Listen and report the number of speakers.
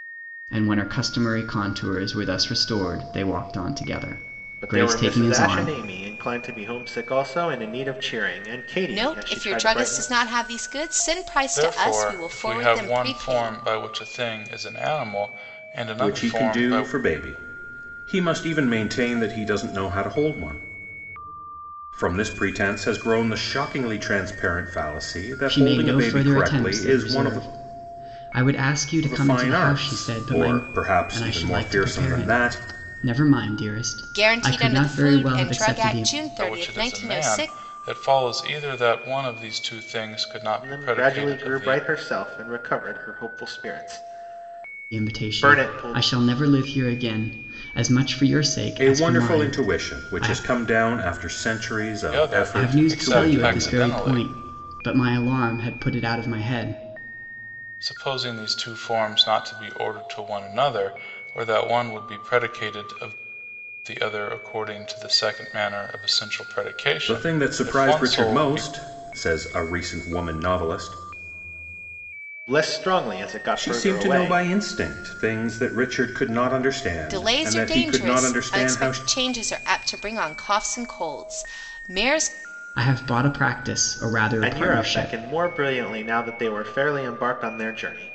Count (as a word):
five